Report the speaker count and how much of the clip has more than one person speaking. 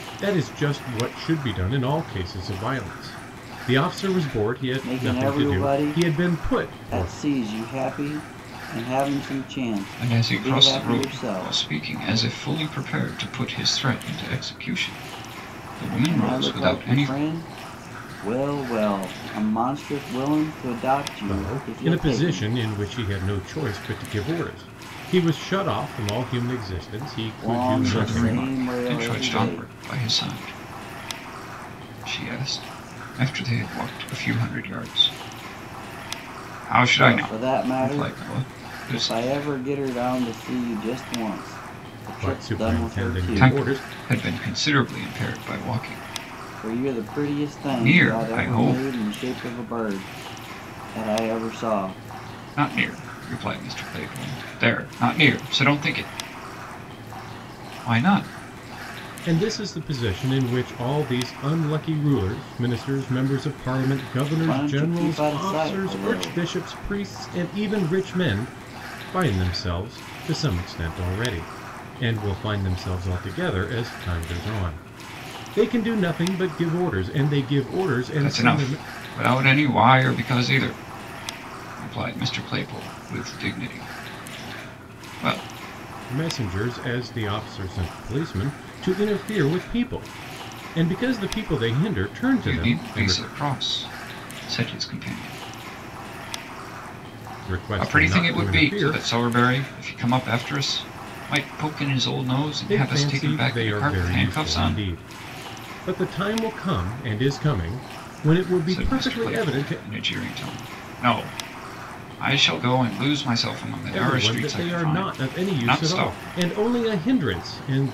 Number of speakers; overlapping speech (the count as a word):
three, about 22%